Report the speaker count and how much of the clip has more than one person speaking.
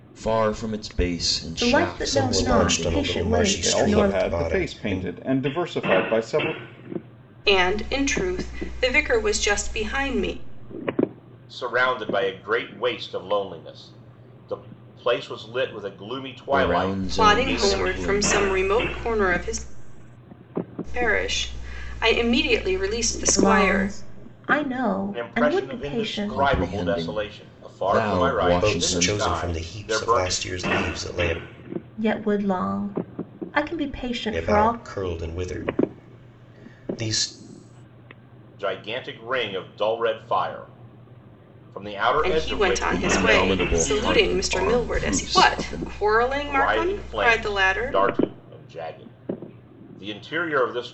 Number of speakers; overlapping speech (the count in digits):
6, about 33%